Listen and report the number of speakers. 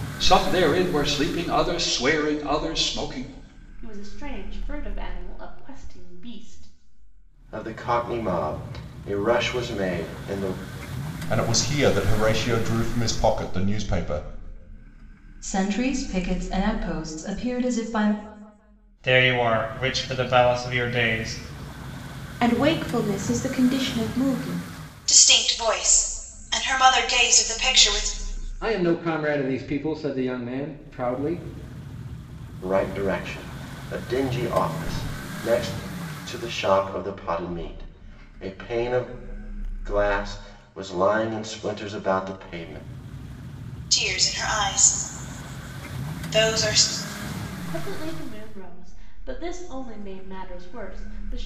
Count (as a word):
nine